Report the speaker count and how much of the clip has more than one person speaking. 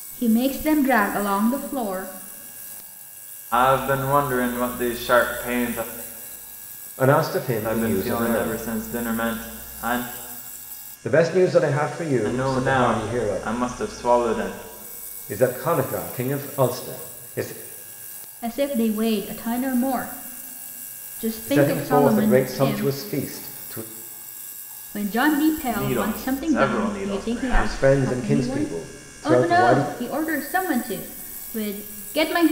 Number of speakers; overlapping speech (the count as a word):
three, about 24%